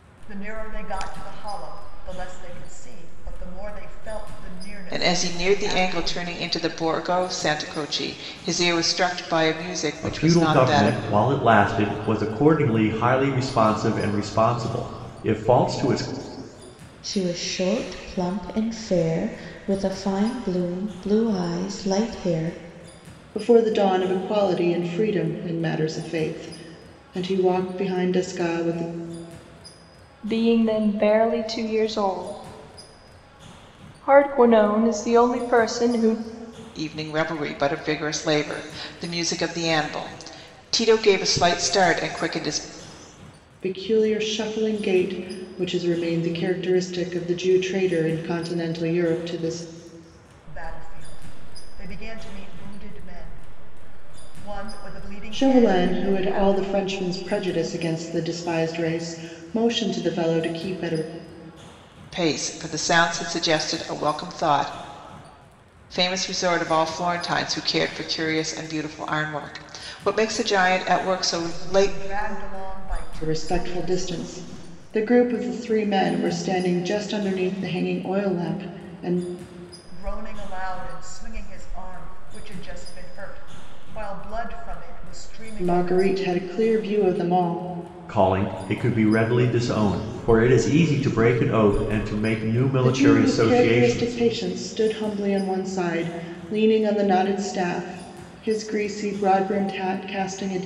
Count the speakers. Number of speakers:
six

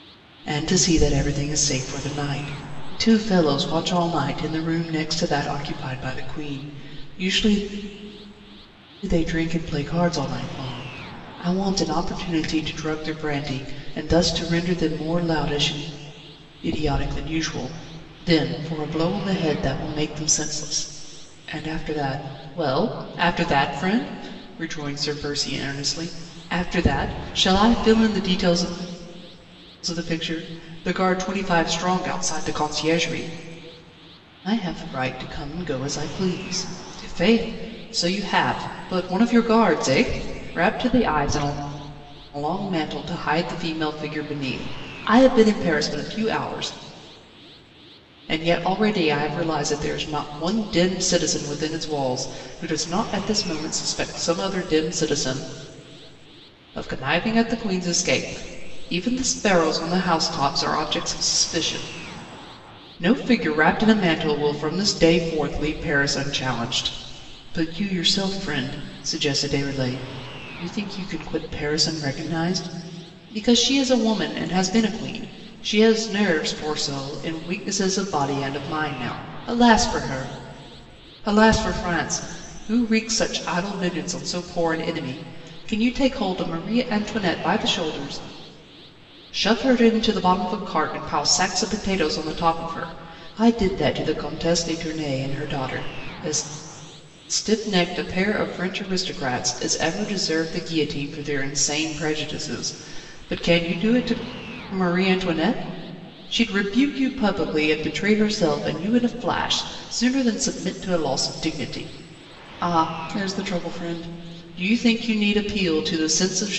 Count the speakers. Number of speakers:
one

